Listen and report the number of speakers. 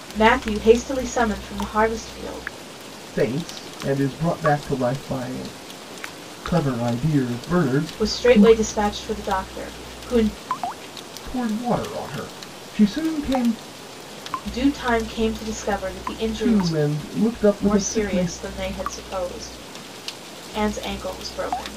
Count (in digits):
2